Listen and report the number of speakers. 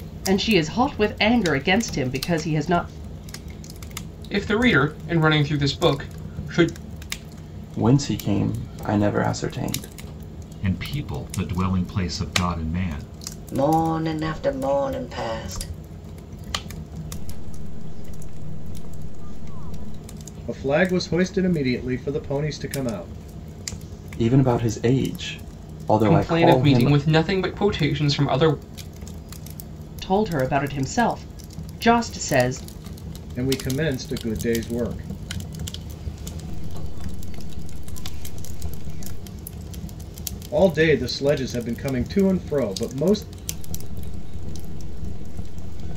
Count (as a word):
seven